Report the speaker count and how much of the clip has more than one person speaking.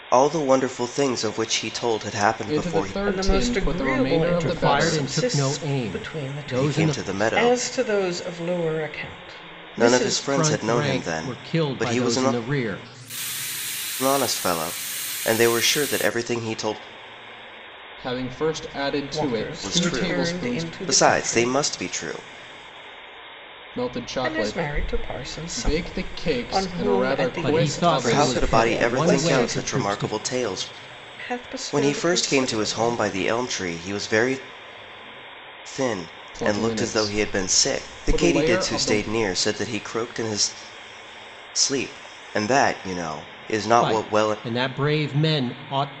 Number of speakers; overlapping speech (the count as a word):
four, about 46%